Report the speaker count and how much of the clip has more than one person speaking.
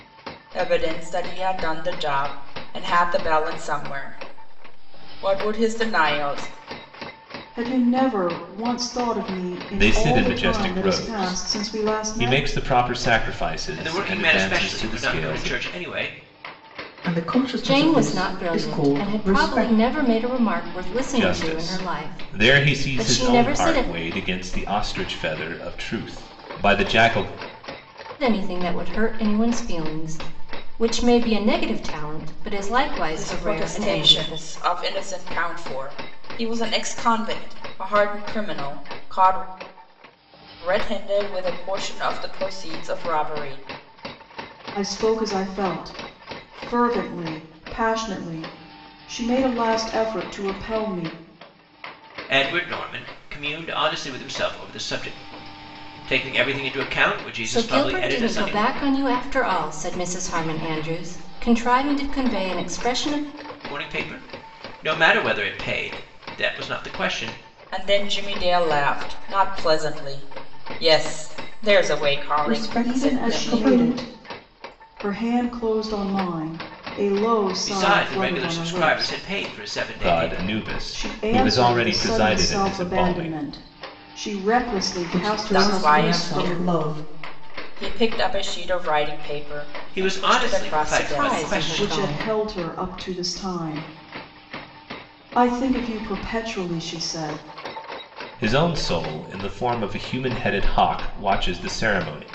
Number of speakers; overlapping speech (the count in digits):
6, about 23%